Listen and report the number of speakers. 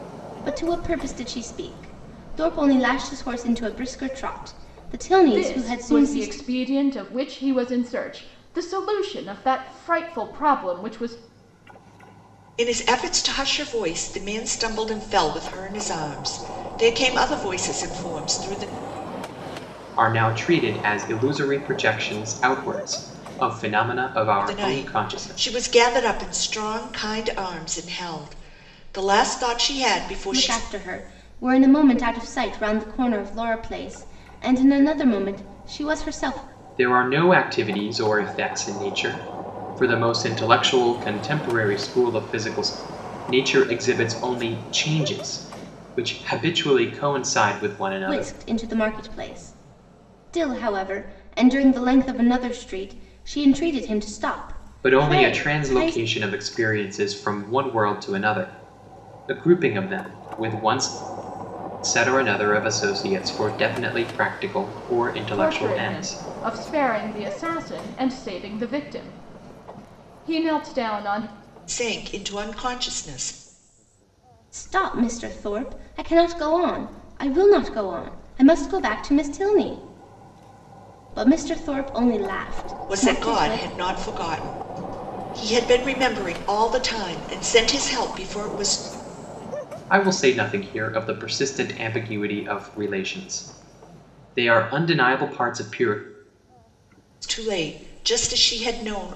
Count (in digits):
4